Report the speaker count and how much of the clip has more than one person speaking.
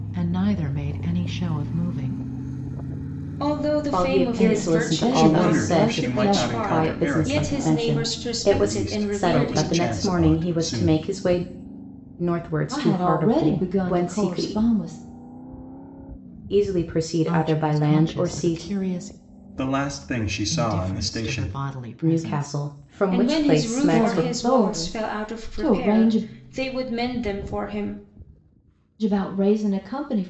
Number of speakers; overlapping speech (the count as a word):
five, about 51%